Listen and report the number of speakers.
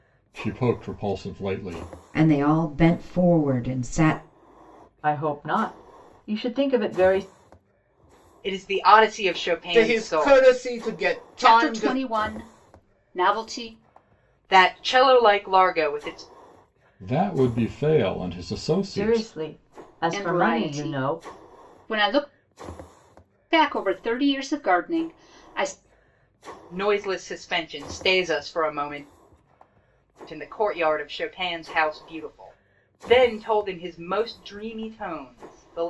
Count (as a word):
six